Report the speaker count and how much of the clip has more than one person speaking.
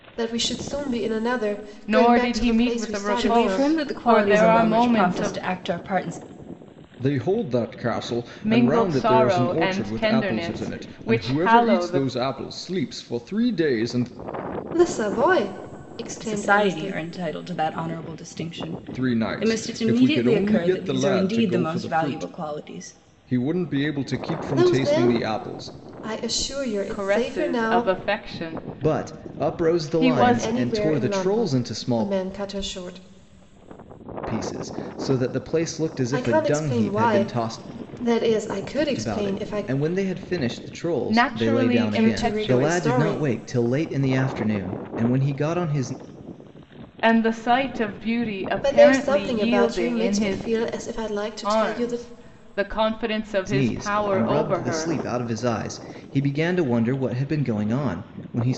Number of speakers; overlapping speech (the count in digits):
4, about 44%